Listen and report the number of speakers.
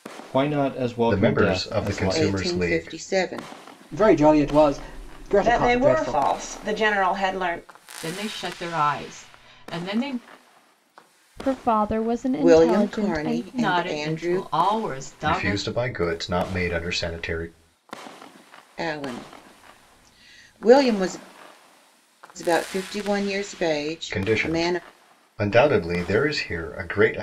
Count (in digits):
7